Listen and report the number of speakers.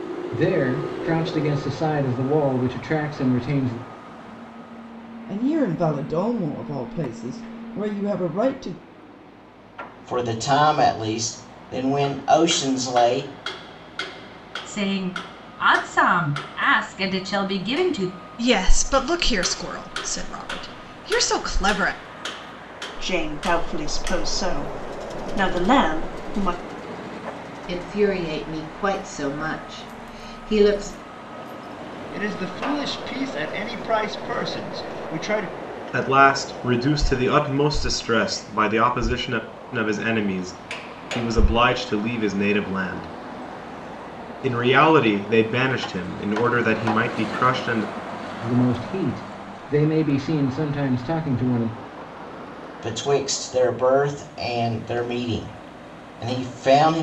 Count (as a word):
nine